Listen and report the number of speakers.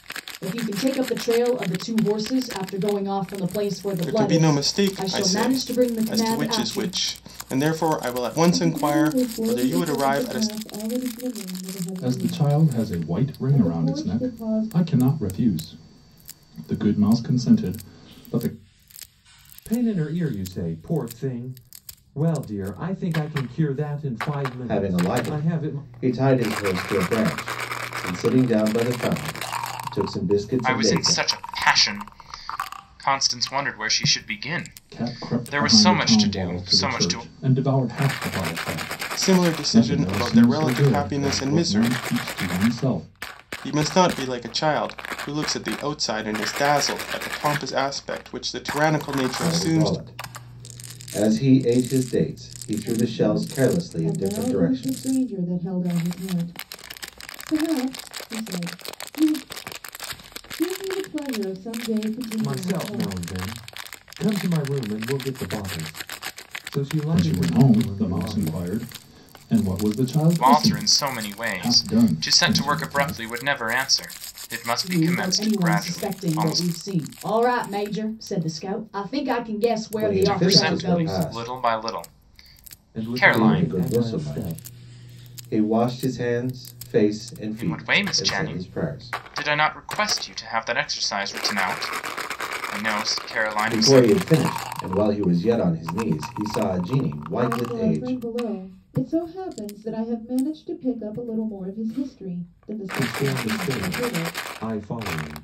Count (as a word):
seven